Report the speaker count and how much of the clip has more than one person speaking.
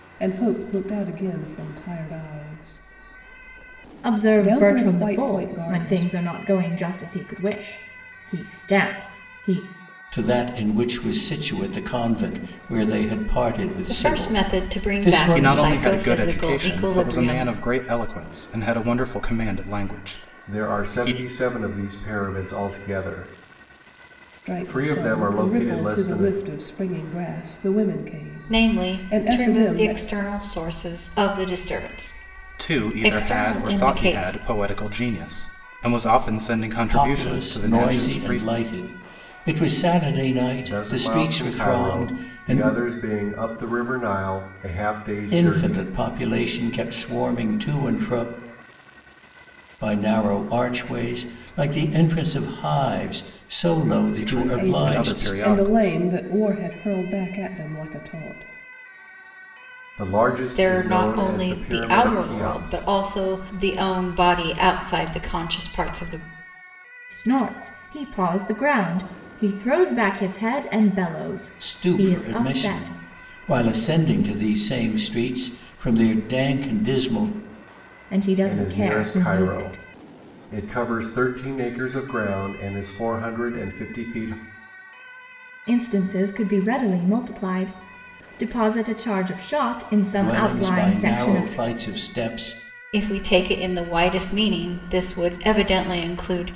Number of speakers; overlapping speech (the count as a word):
six, about 25%